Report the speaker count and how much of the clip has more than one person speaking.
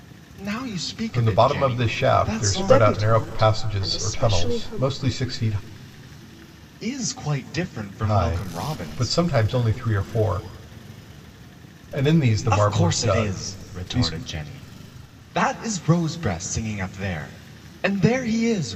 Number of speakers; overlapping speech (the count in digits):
3, about 36%